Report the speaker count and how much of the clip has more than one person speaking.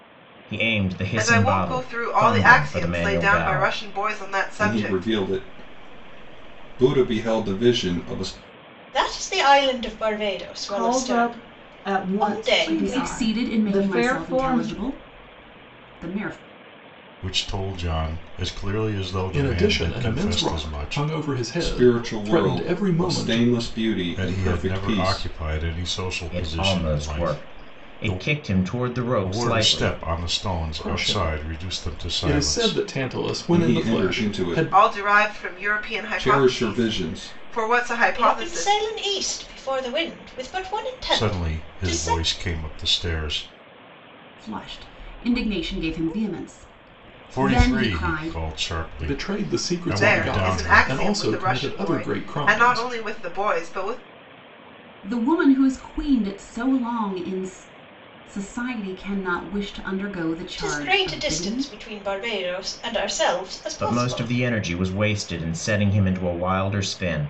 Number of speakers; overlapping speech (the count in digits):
8, about 44%